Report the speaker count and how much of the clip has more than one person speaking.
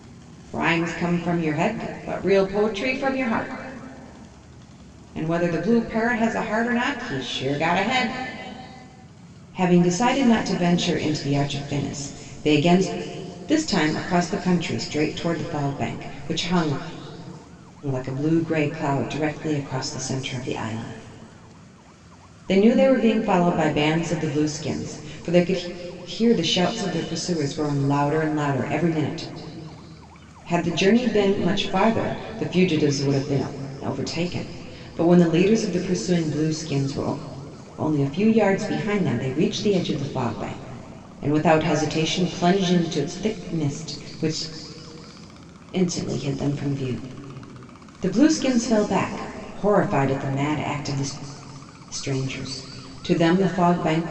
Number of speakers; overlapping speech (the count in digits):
1, no overlap